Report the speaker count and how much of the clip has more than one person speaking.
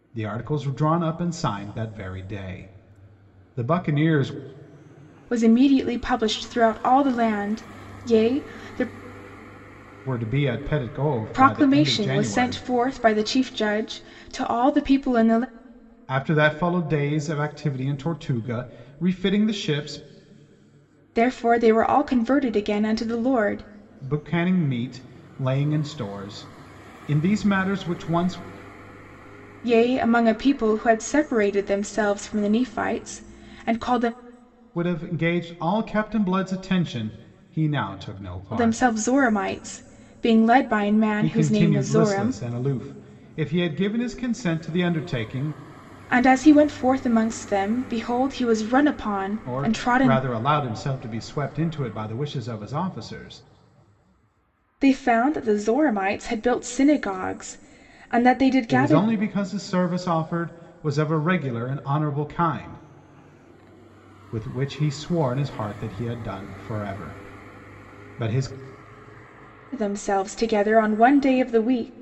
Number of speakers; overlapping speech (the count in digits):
2, about 6%